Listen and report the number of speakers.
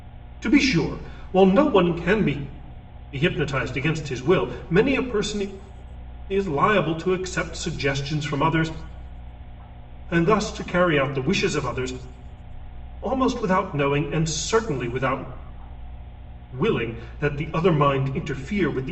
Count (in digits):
1